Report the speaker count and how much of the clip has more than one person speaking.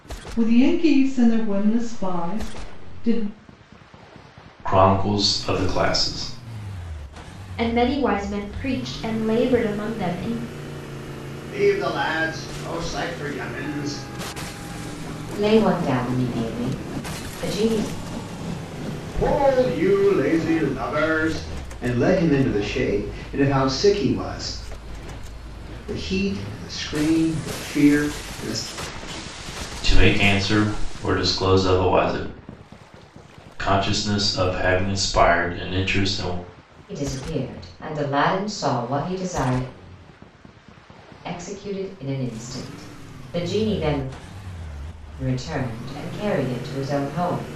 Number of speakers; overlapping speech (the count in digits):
5, no overlap